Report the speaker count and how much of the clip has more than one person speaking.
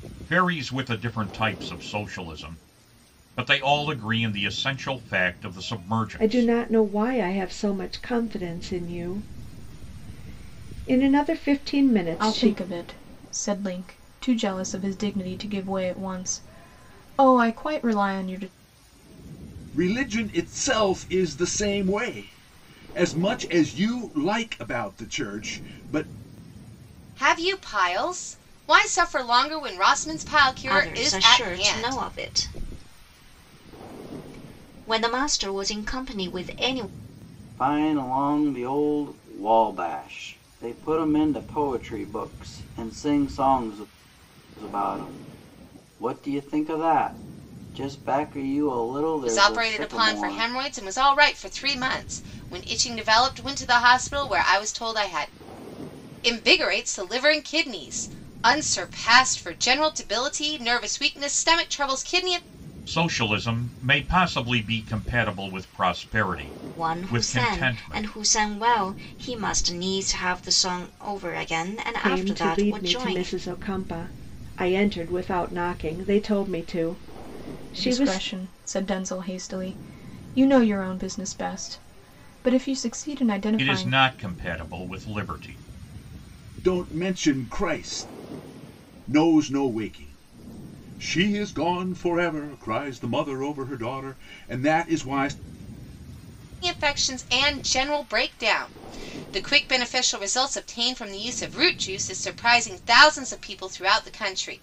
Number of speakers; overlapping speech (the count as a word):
seven, about 7%